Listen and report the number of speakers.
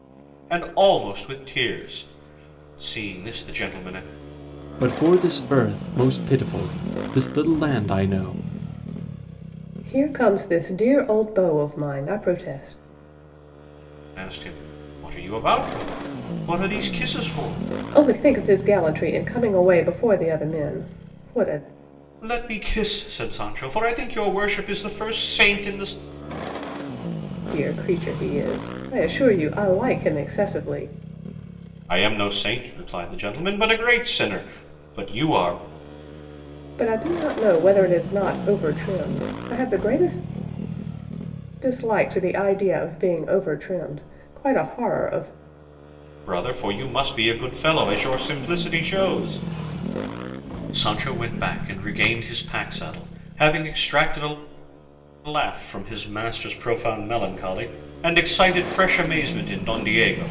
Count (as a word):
three